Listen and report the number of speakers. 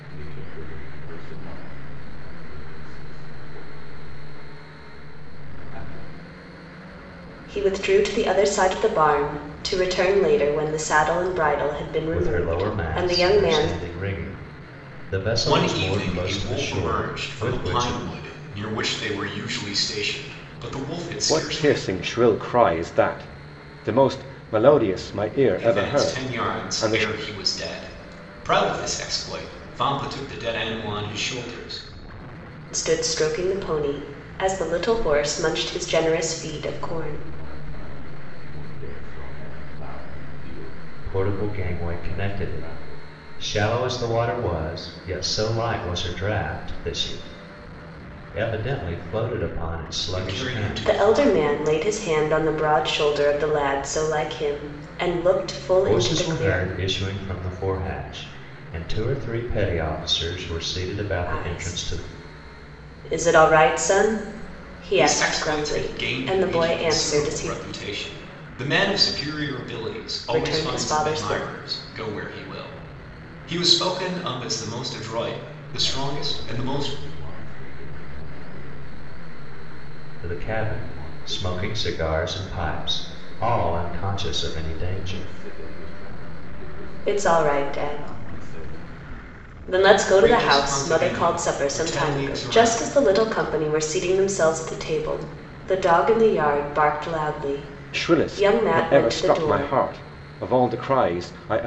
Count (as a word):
five